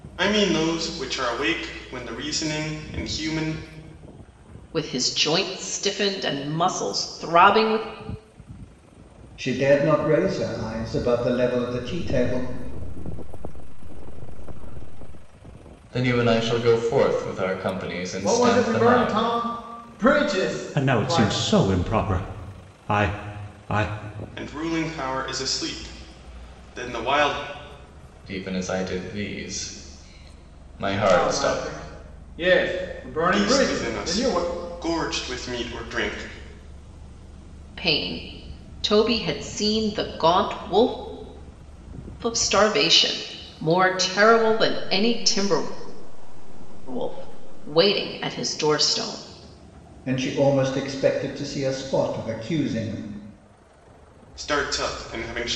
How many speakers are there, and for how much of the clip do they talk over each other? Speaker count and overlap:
7, about 12%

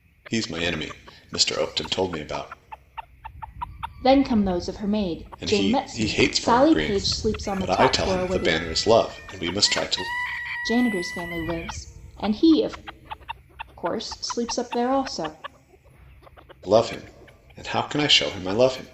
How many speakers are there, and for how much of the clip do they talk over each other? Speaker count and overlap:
2, about 16%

